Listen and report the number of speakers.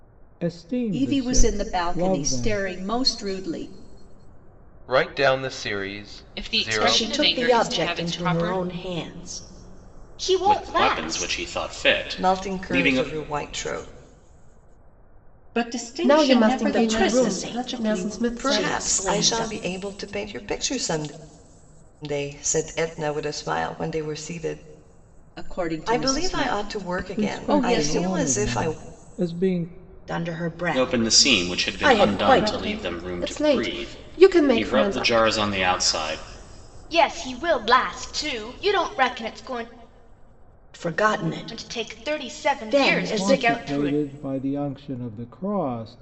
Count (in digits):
10